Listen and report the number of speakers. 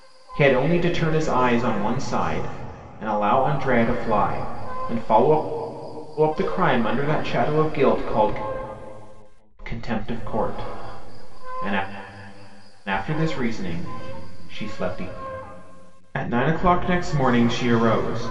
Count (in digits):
1